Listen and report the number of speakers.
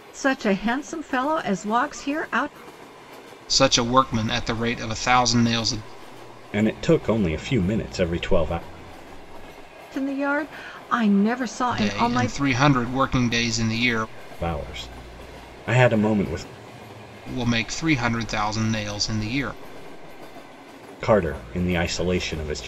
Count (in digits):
3